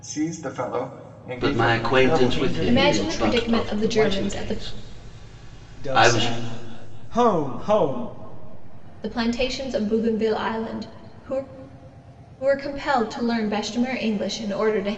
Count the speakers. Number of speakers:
4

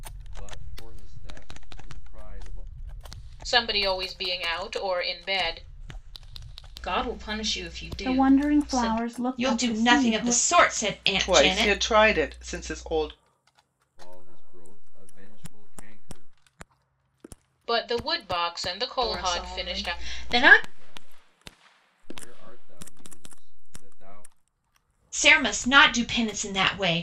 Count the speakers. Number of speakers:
6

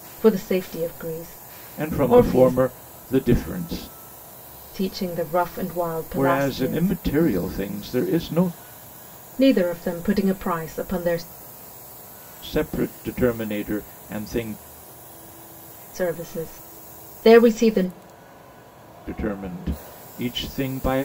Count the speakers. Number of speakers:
2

